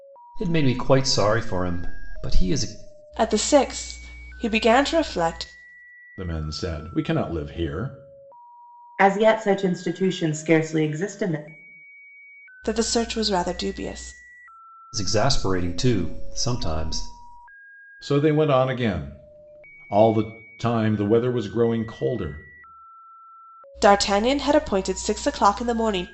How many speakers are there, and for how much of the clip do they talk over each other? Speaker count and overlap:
four, no overlap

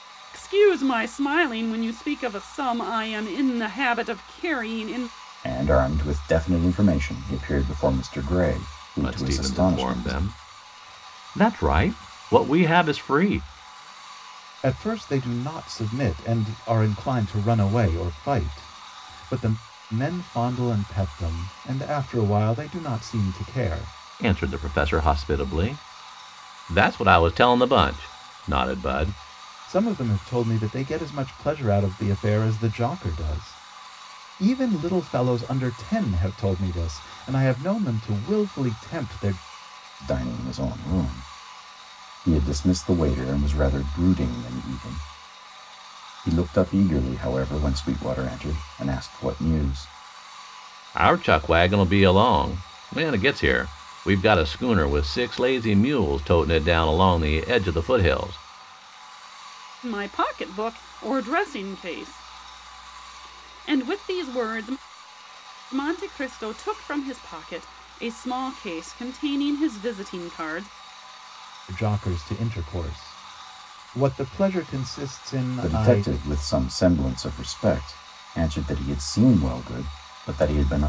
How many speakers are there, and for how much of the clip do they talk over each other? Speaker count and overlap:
four, about 2%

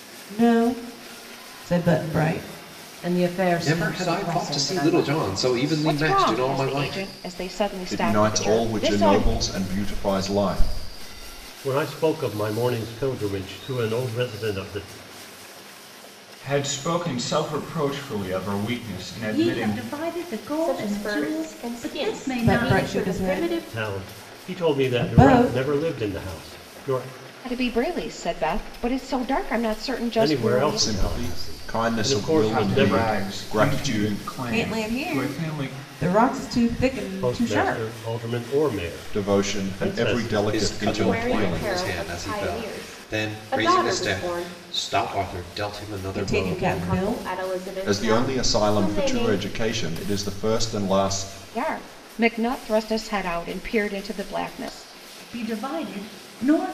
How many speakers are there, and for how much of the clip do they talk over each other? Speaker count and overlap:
nine, about 44%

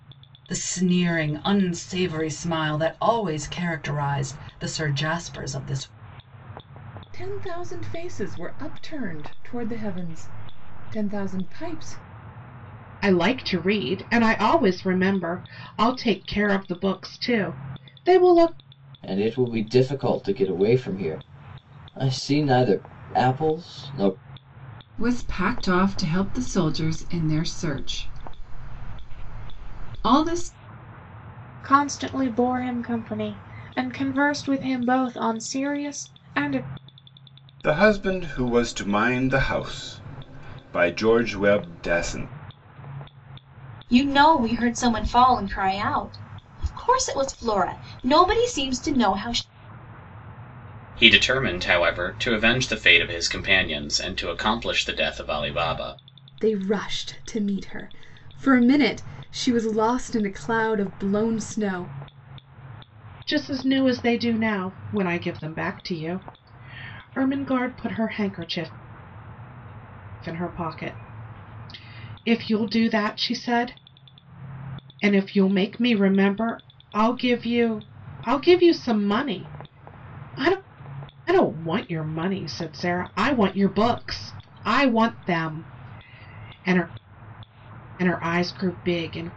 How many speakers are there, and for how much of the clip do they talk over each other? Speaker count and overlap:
ten, no overlap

